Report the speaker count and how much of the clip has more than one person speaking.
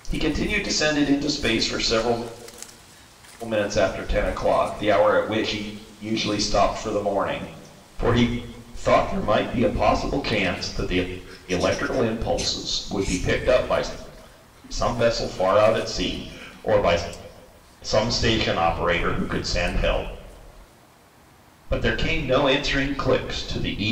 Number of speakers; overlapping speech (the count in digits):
1, no overlap